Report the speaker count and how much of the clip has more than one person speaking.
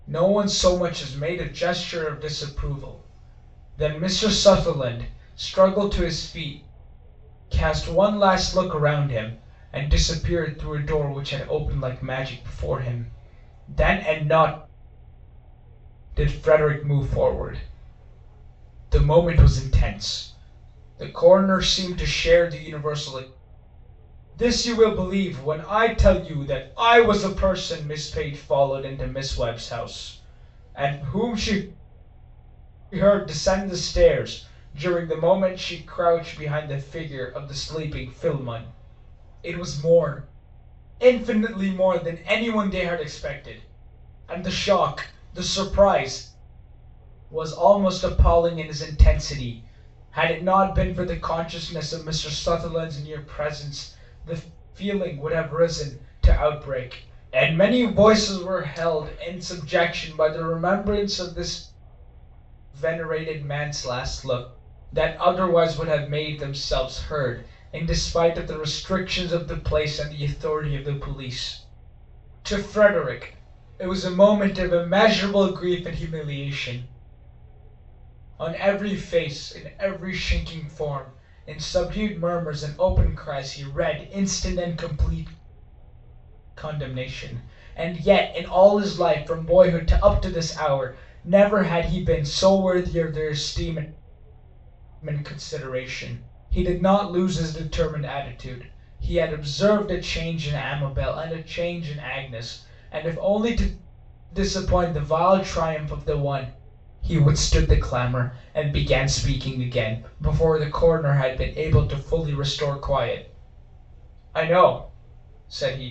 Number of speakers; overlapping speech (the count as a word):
one, no overlap